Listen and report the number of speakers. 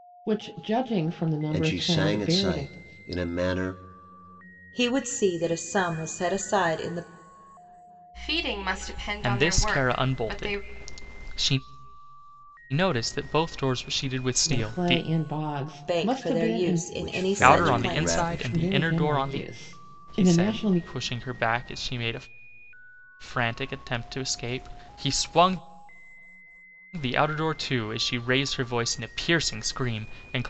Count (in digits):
5